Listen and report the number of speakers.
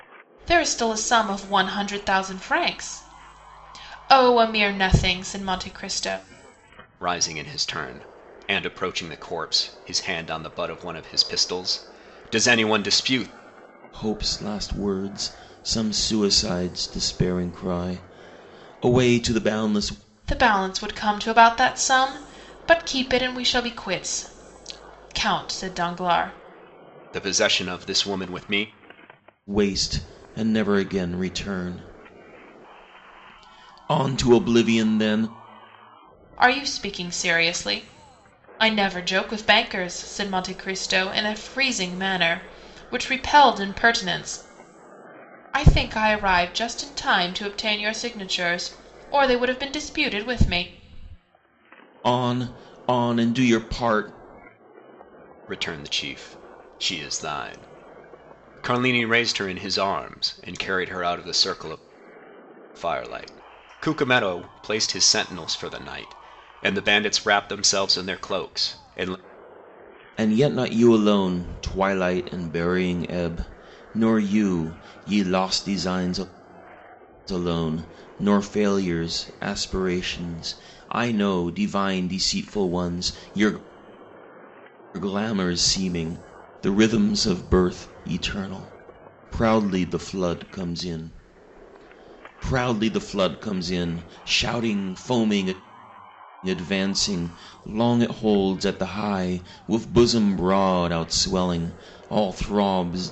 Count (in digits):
3